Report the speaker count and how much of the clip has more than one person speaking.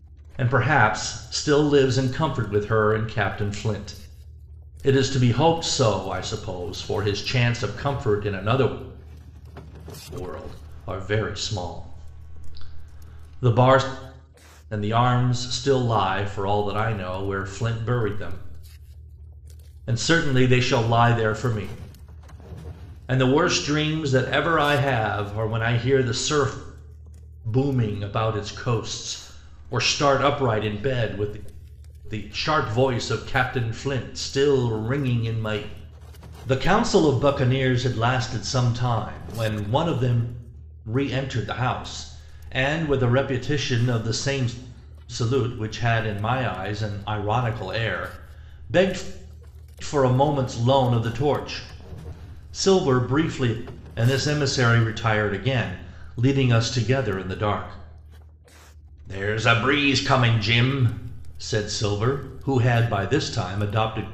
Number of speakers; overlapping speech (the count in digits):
1, no overlap